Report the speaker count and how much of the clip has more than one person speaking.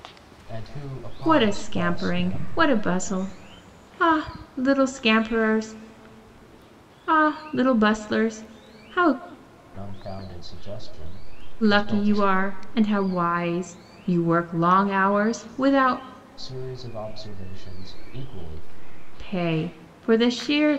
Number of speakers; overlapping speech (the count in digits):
2, about 9%